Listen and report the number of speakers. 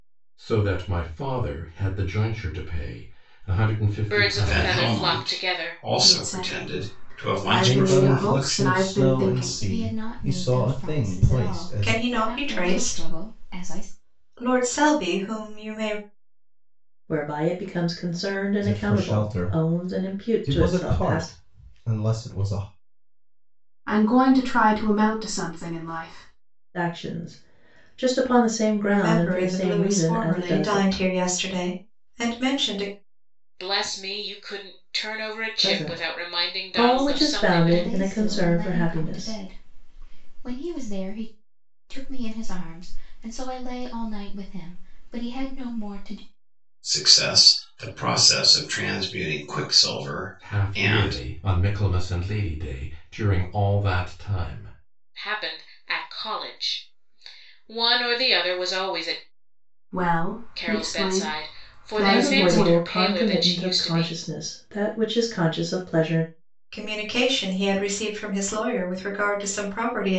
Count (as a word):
eight